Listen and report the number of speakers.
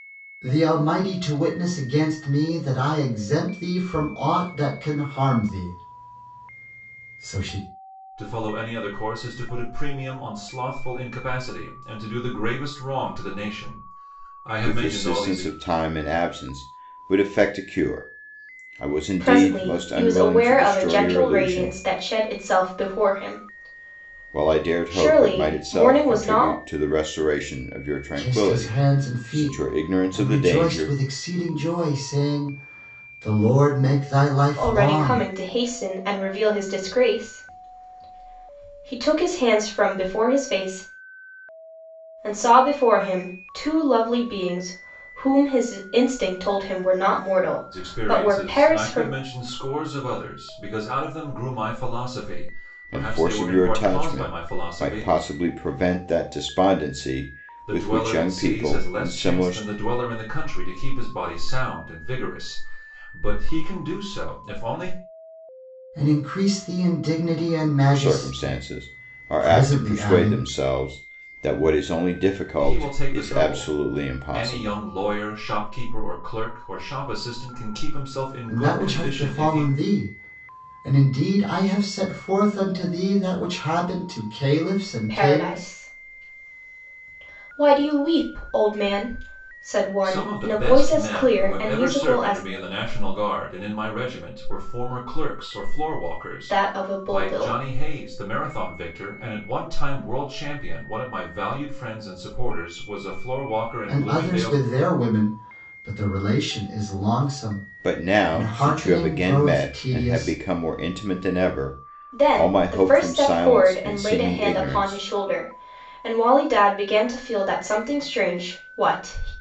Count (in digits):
4